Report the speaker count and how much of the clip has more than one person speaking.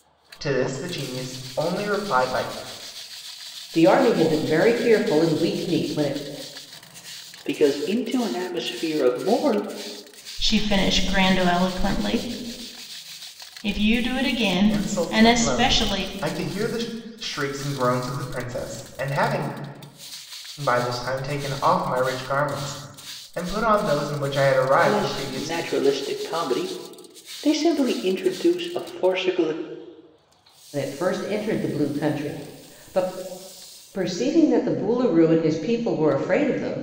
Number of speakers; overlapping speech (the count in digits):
4, about 6%